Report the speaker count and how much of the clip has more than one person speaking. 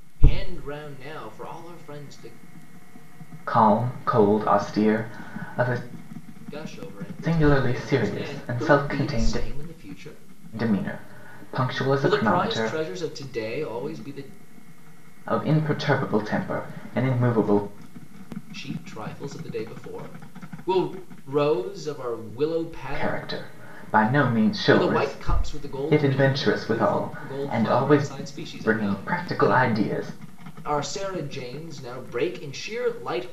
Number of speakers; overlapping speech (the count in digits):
2, about 22%